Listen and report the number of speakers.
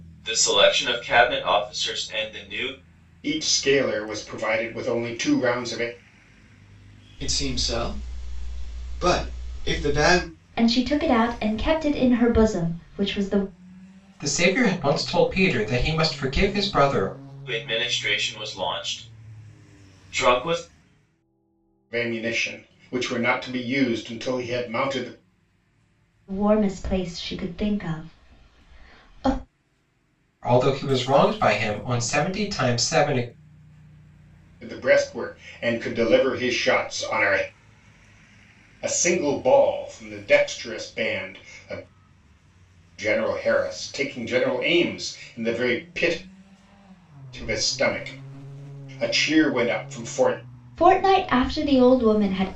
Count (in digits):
5